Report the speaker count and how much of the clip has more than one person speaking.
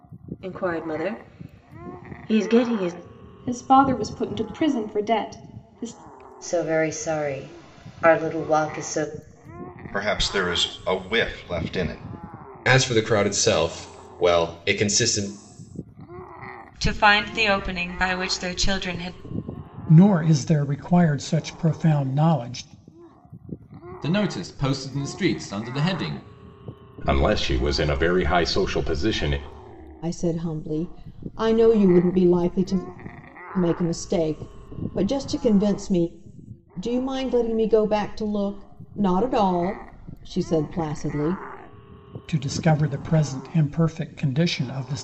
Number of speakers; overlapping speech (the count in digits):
10, no overlap